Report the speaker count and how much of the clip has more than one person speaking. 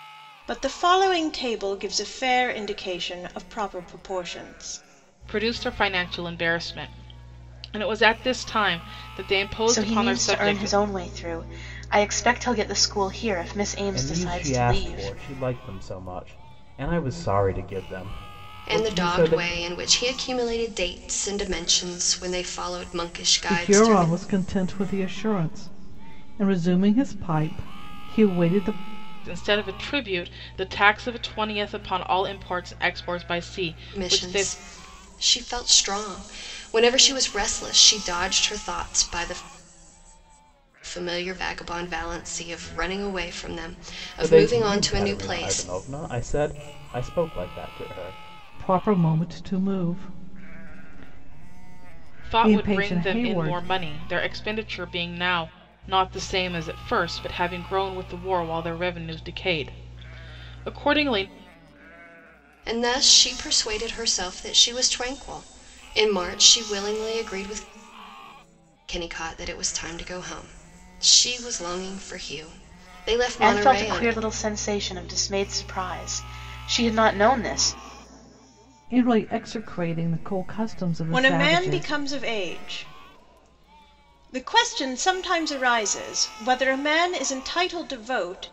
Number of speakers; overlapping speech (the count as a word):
six, about 10%